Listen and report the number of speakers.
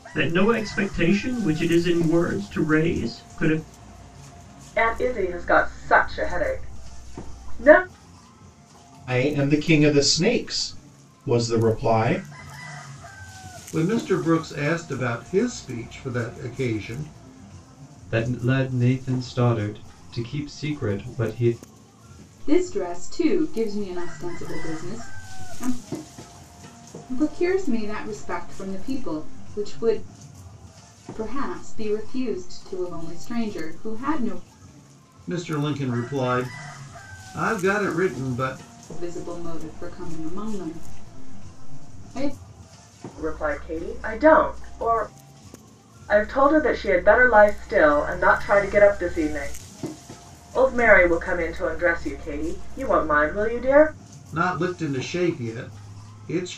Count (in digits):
6